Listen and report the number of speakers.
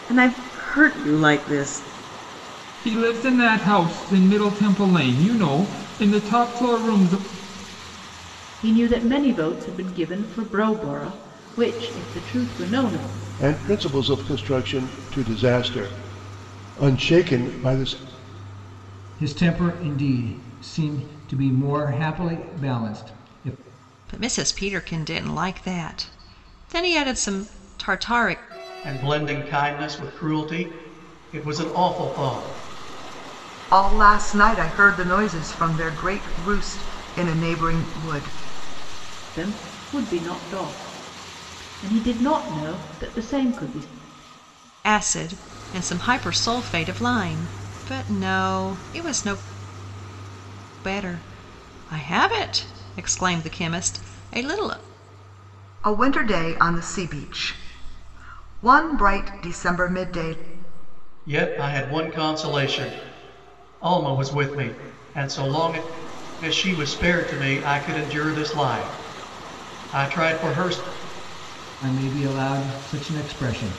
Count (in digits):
8